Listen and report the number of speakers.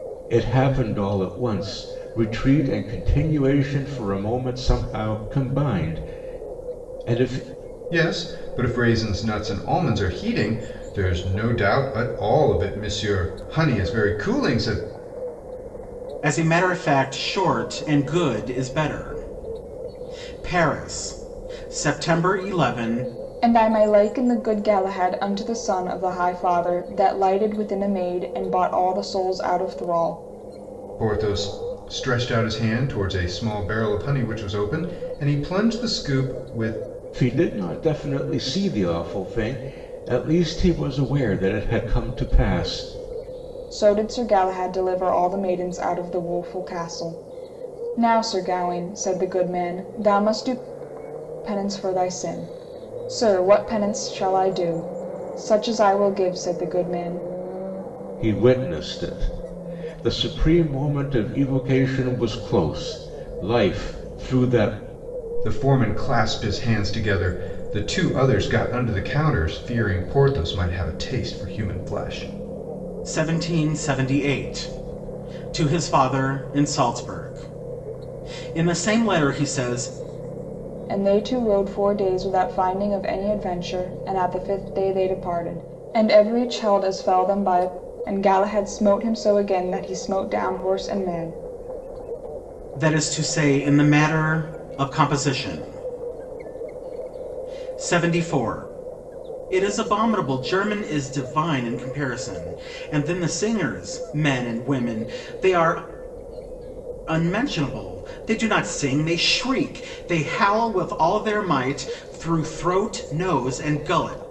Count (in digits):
4